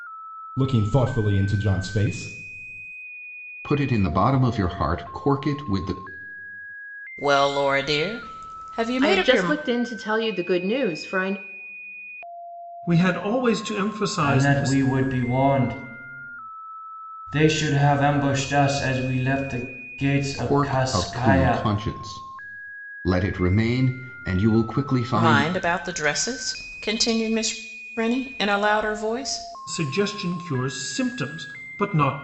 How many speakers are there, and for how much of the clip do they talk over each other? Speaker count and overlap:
6, about 9%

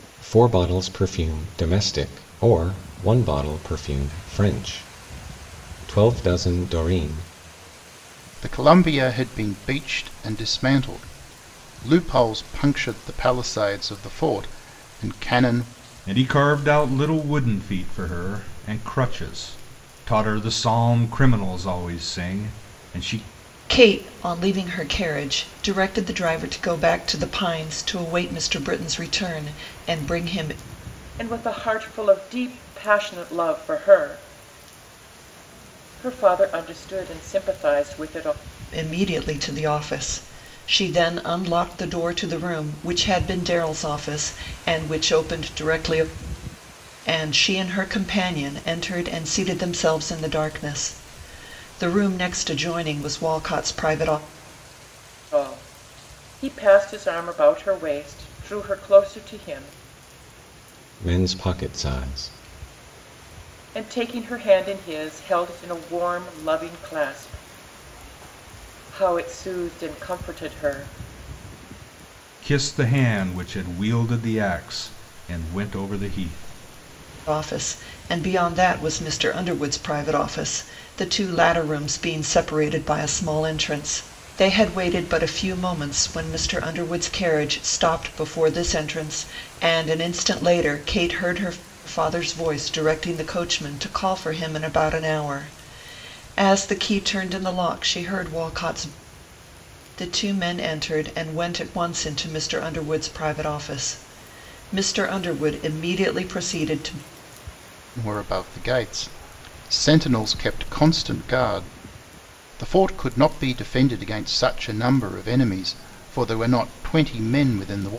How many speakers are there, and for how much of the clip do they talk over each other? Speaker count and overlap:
5, no overlap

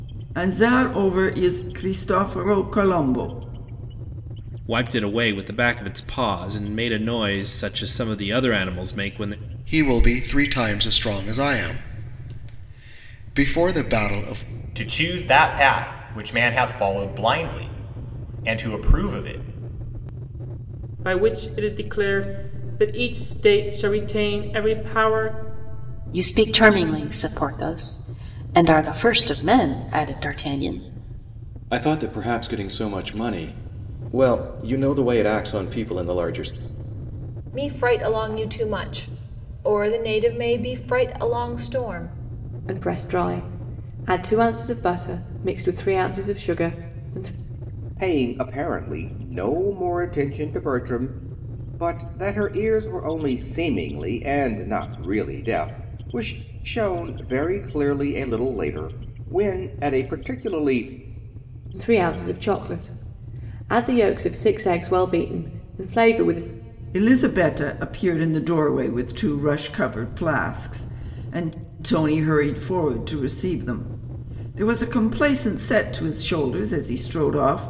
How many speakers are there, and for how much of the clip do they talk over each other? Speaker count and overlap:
10, no overlap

